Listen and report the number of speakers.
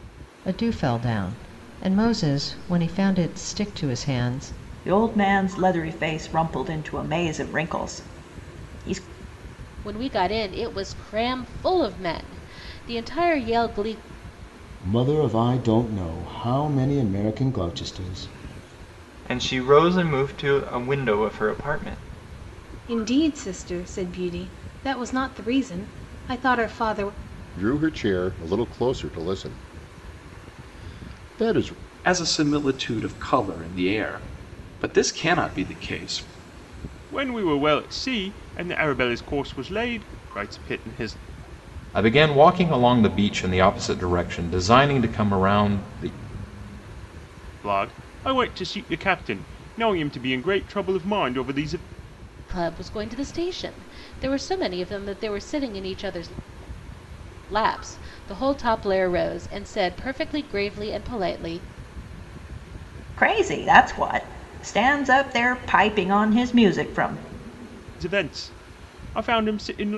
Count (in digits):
10